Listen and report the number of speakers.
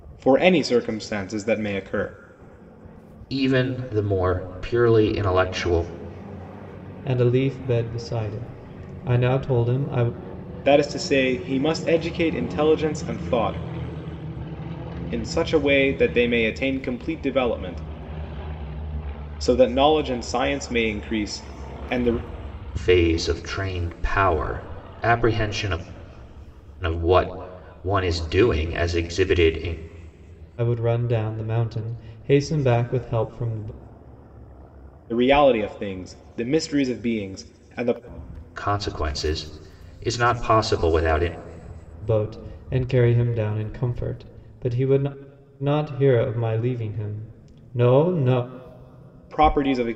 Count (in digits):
3